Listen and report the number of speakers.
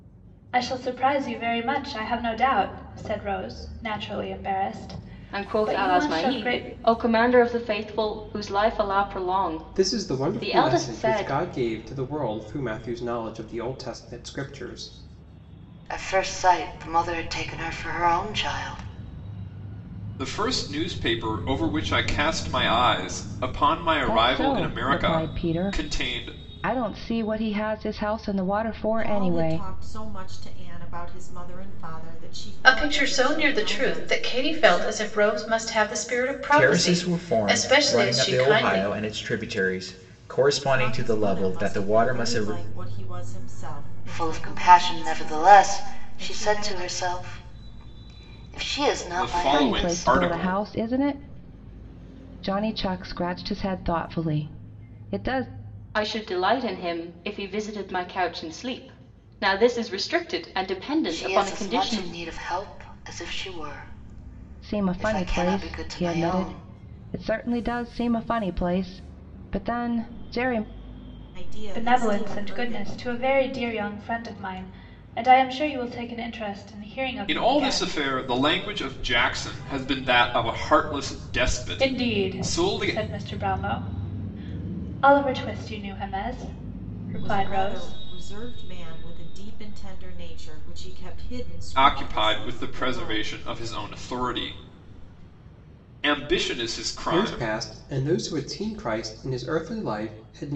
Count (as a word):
nine